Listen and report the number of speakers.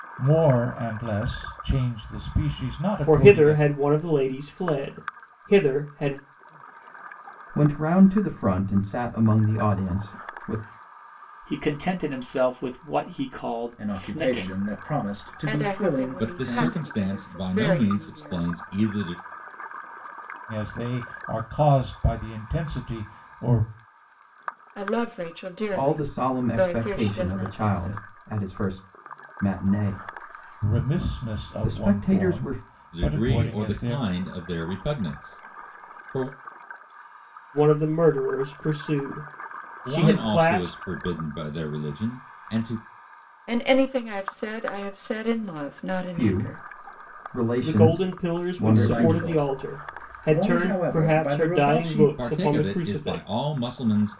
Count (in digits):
7